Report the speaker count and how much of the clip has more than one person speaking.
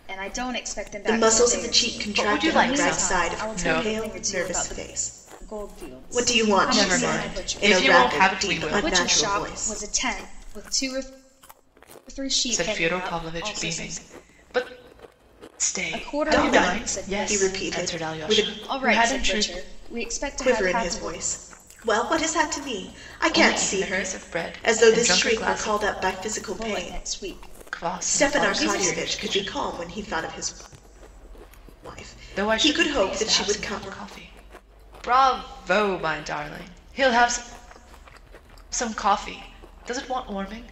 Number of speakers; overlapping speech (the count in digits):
3, about 48%